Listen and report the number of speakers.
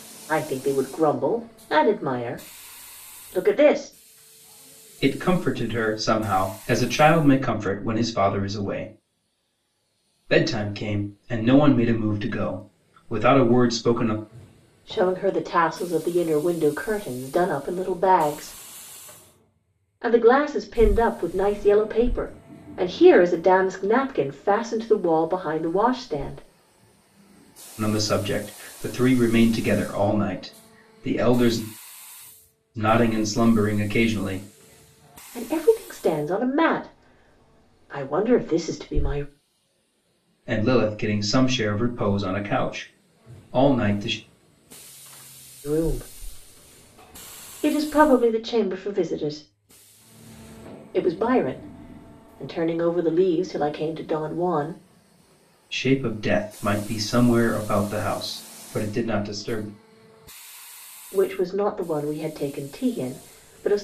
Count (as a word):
two